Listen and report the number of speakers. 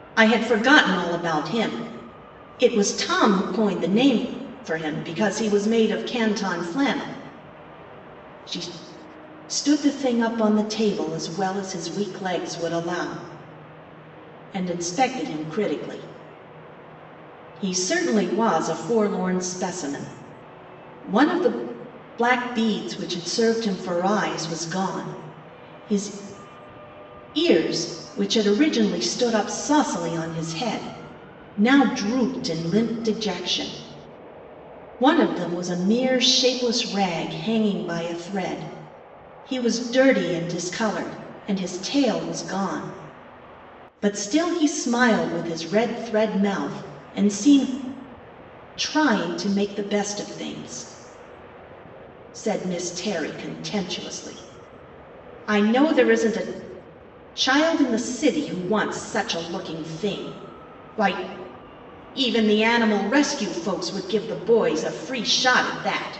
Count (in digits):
1